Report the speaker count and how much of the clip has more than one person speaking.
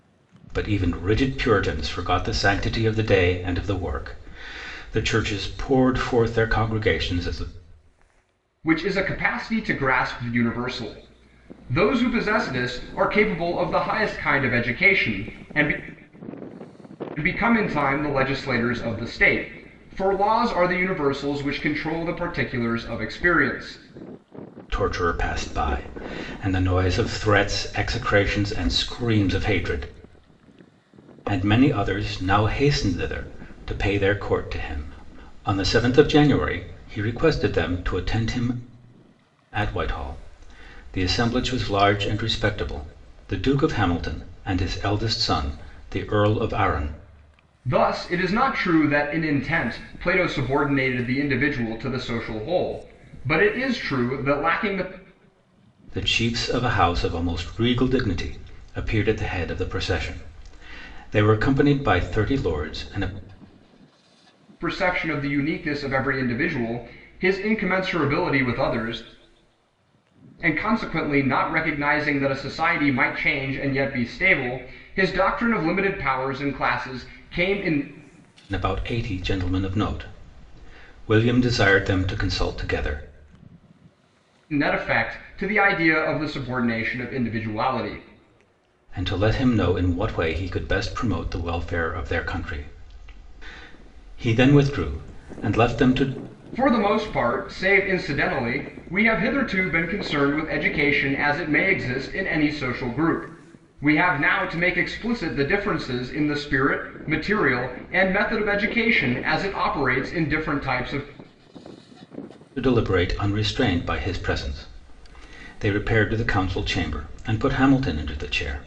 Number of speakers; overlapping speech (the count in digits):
2, no overlap